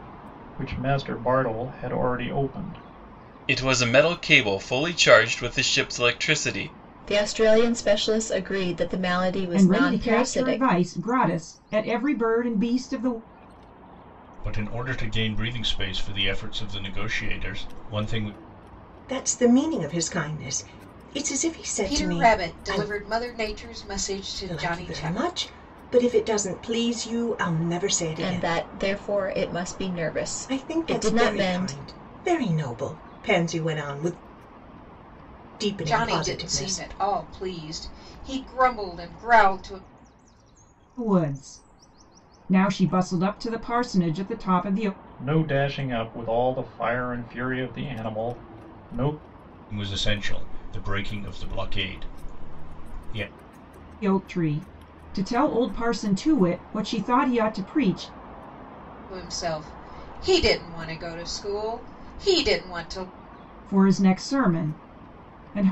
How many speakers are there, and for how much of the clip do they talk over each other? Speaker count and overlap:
seven, about 9%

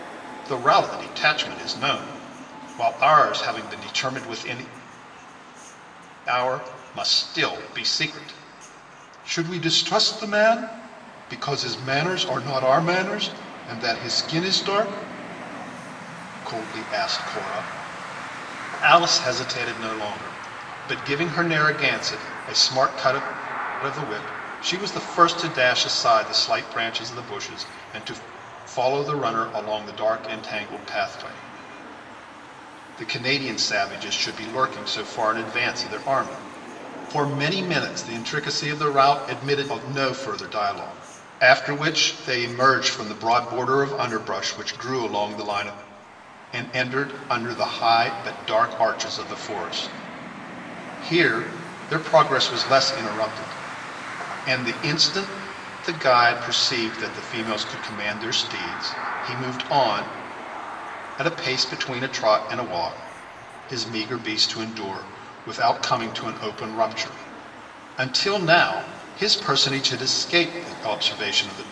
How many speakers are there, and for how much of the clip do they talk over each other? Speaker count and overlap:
one, no overlap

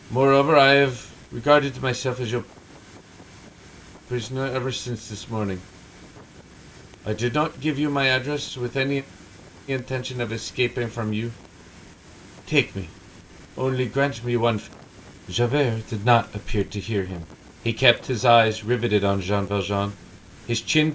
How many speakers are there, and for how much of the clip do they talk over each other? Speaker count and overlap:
one, no overlap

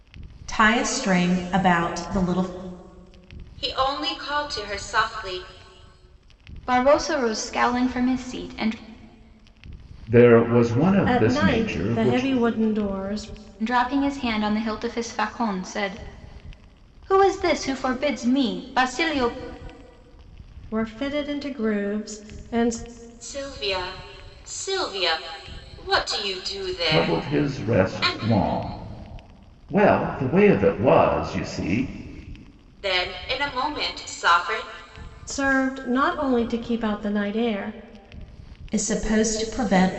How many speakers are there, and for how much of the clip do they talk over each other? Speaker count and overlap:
five, about 7%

